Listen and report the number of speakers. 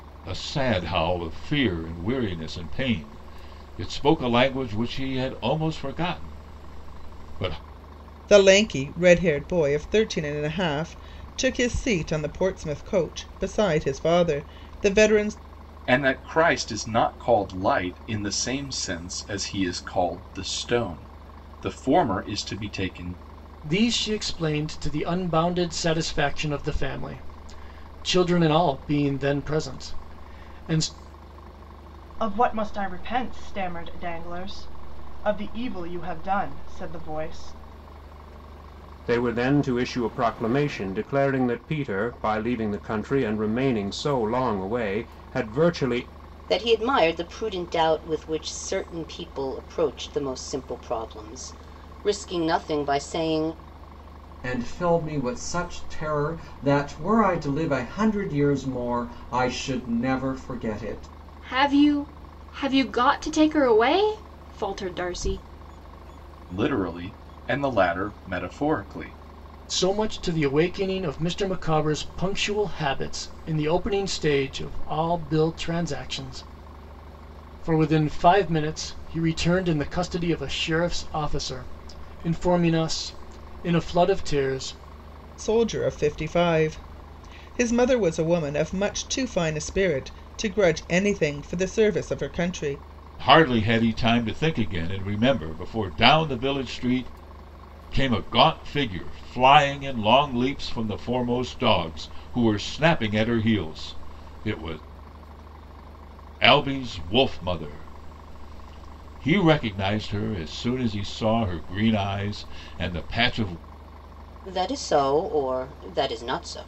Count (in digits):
9